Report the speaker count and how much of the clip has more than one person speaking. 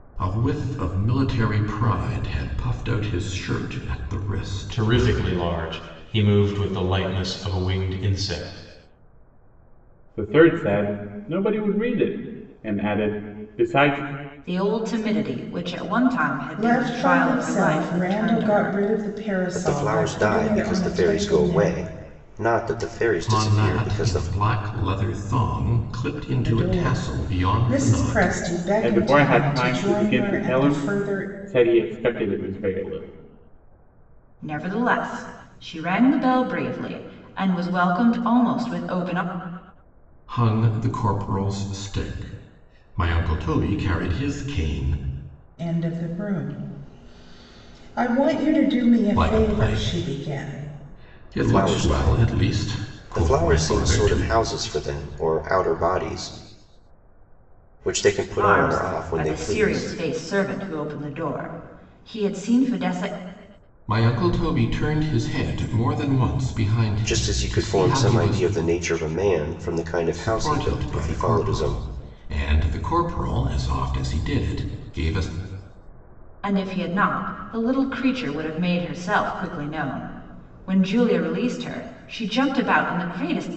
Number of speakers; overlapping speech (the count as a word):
six, about 24%